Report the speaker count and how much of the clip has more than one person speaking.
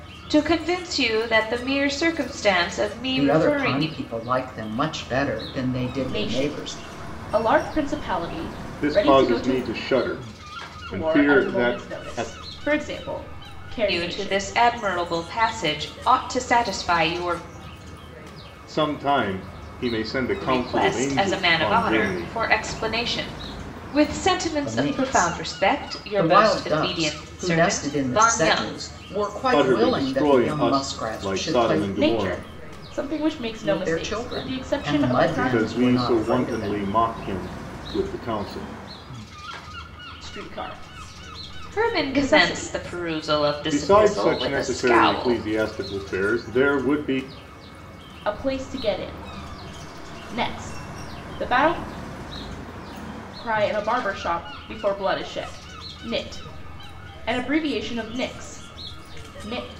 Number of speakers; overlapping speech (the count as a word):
four, about 33%